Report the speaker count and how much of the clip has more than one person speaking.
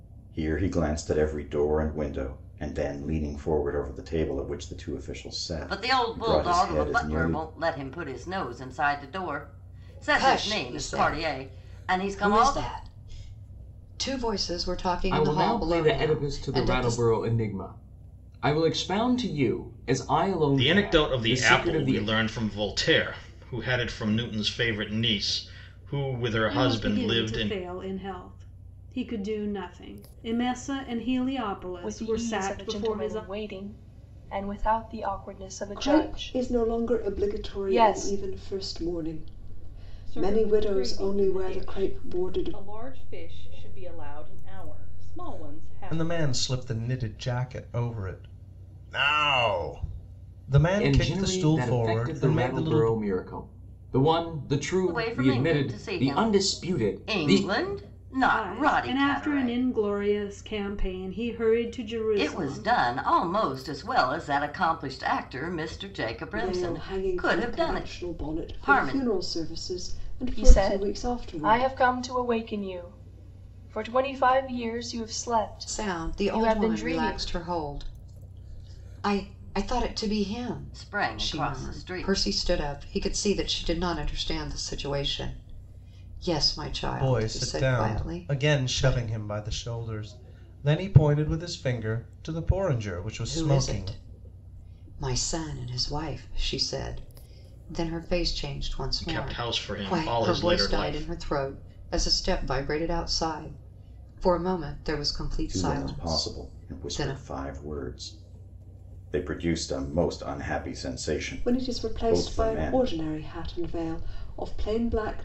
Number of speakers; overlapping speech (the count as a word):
ten, about 33%